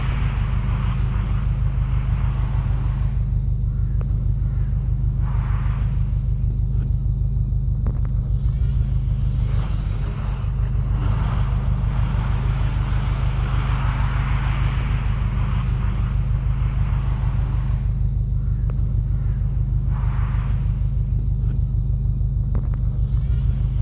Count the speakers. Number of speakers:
zero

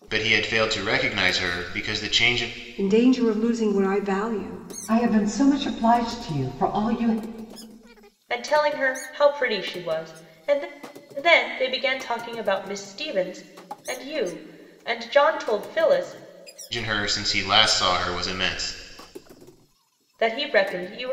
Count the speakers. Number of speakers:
four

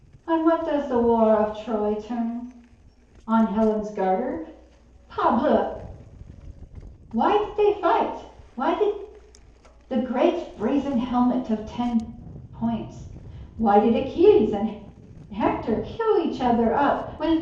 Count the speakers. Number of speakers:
one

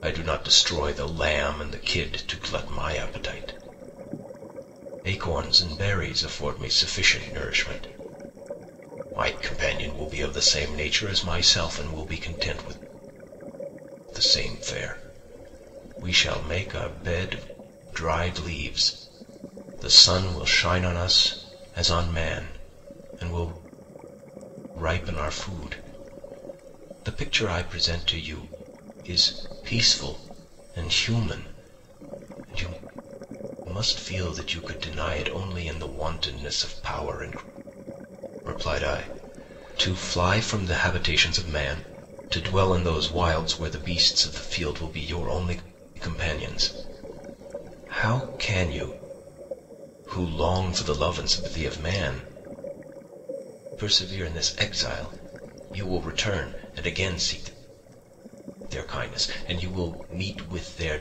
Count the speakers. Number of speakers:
one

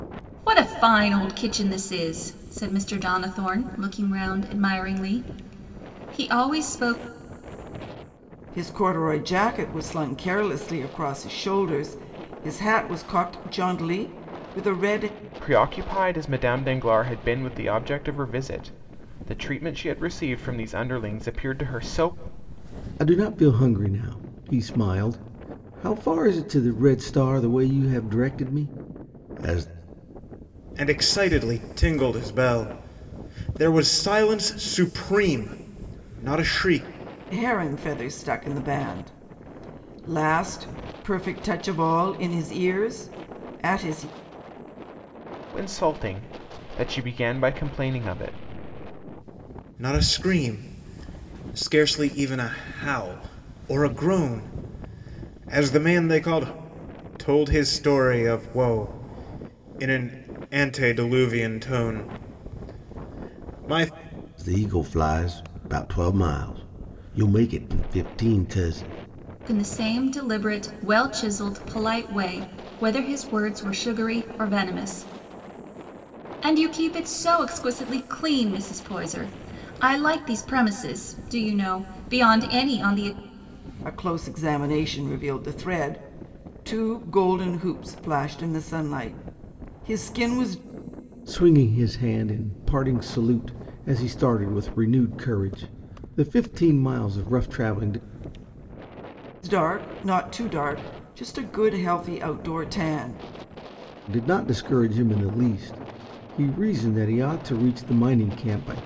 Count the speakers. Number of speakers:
five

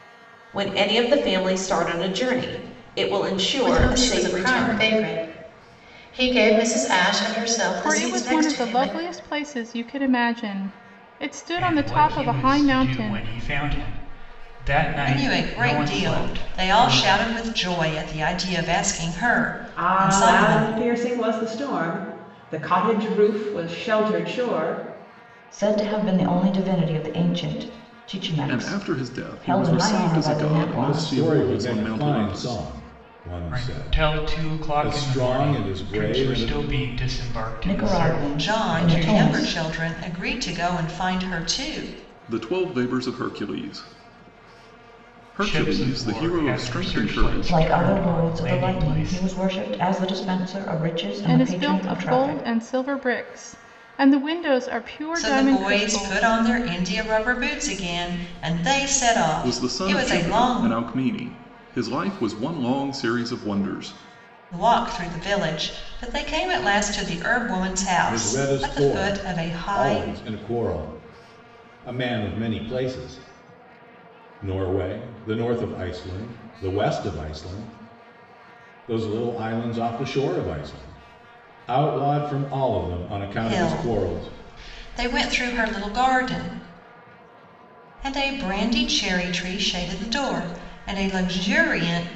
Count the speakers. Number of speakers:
nine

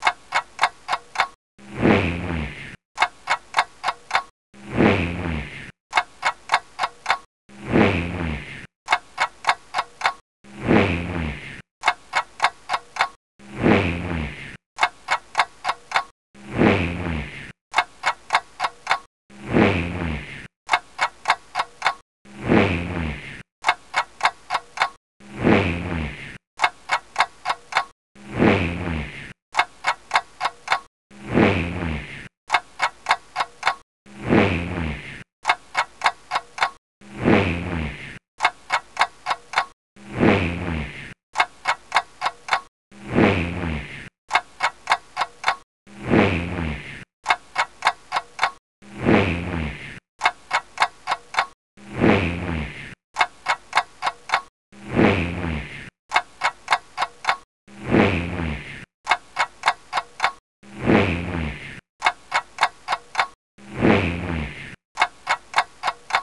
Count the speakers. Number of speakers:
zero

